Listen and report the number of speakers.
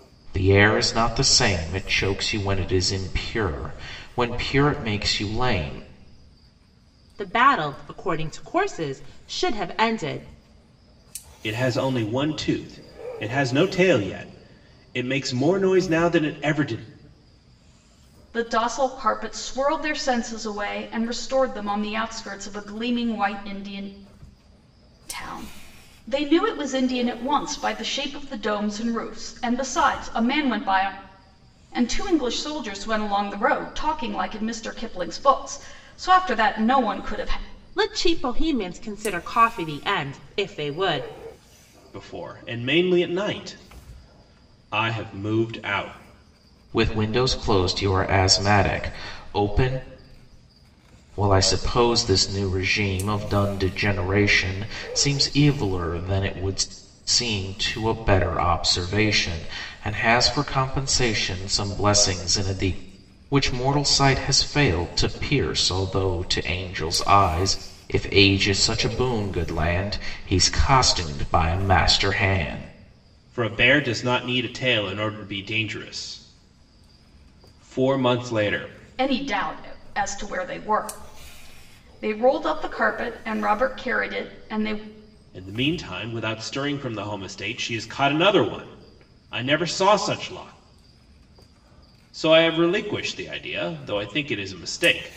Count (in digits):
4